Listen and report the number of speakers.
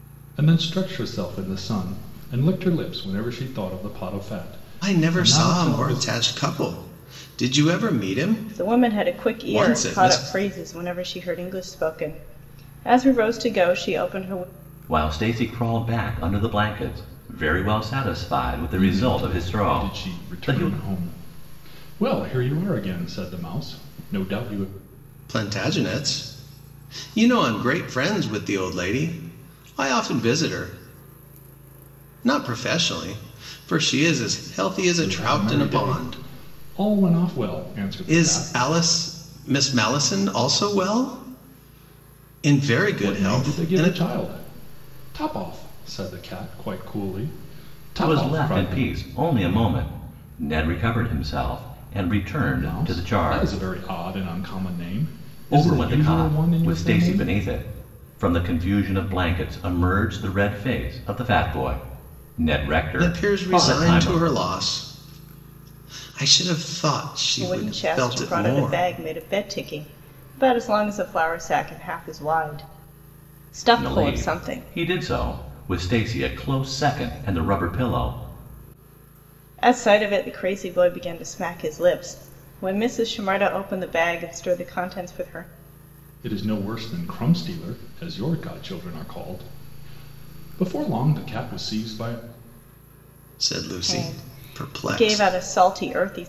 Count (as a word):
four